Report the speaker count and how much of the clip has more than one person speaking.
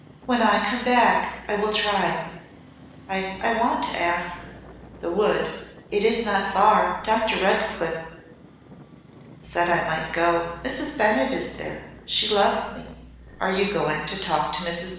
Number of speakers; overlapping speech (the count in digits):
1, no overlap